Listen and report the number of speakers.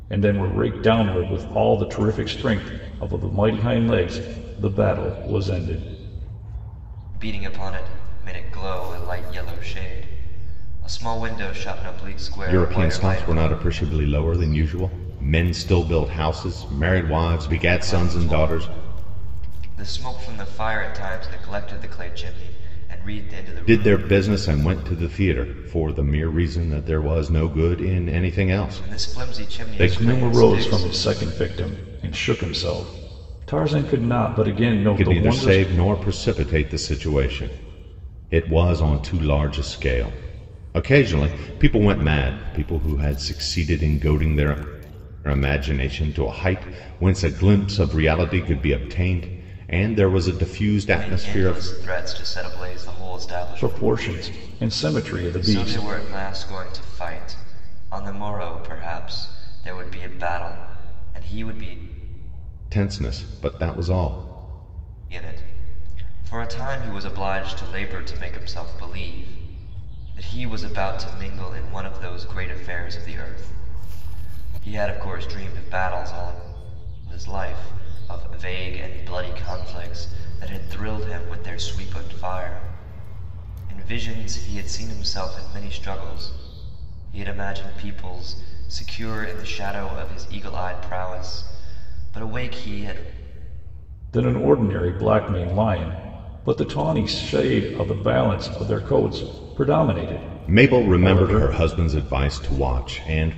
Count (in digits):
3